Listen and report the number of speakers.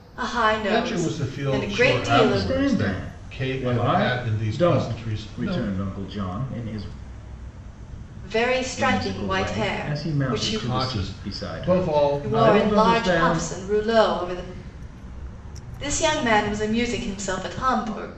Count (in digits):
3